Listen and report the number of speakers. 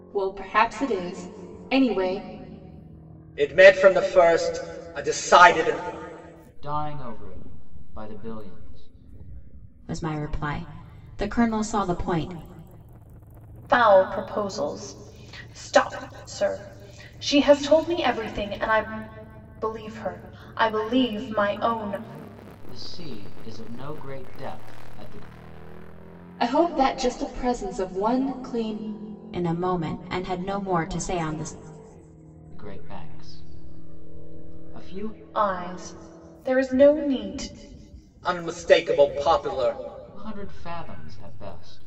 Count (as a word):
five